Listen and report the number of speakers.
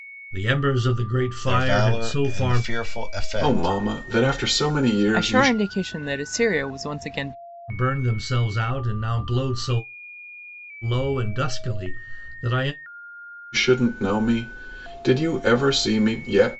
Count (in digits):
4